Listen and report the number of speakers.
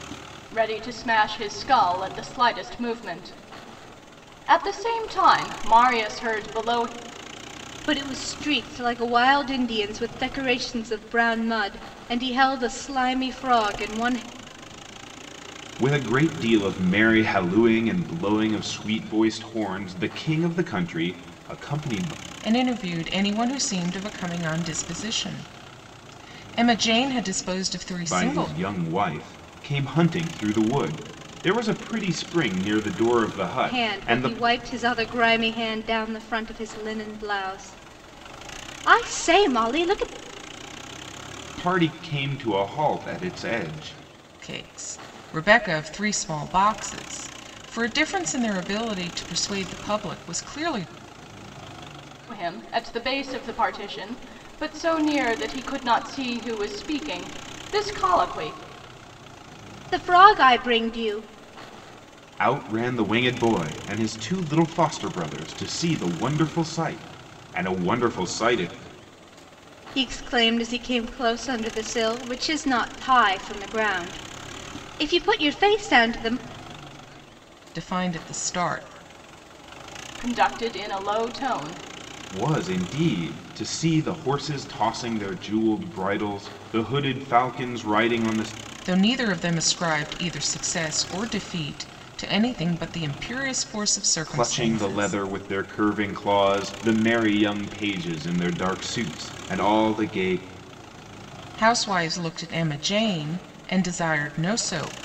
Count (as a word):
four